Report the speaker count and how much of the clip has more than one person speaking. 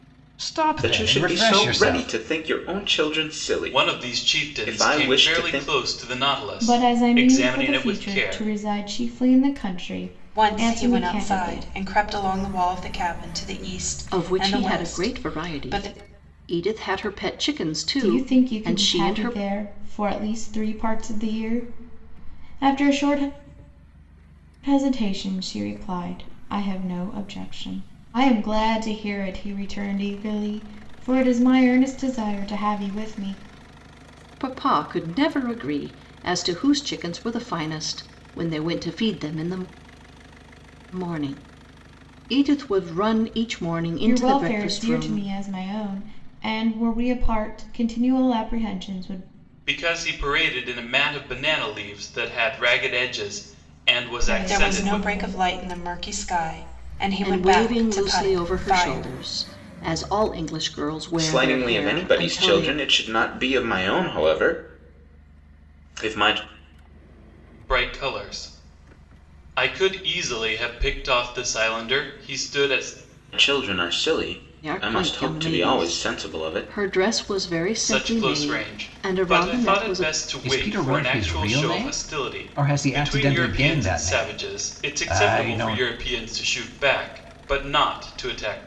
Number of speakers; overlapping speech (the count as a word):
six, about 29%